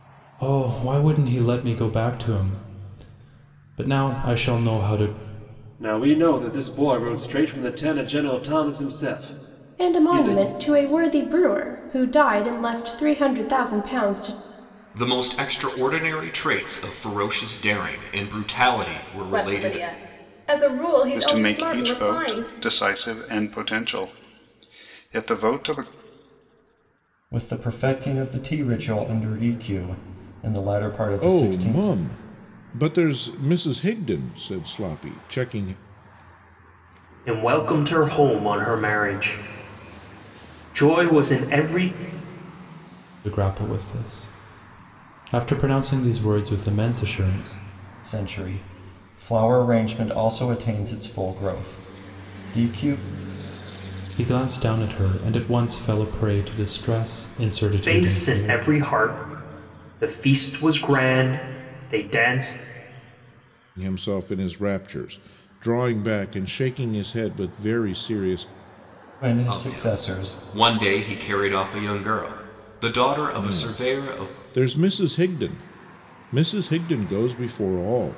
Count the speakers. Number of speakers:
9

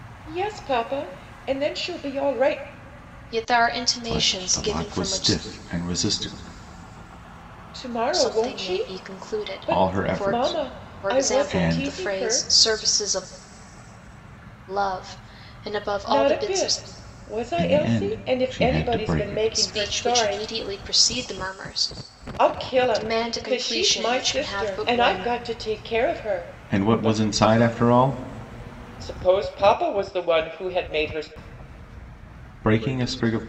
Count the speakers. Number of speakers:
3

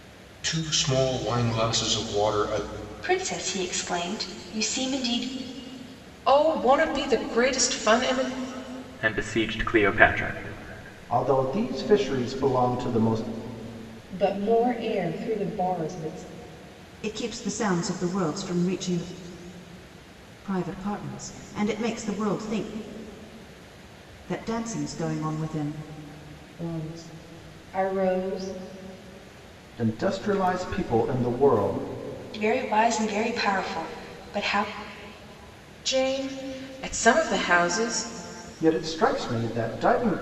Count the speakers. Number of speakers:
7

